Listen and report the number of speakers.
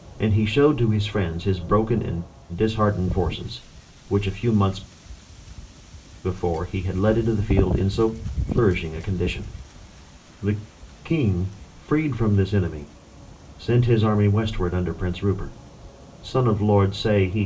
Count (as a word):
one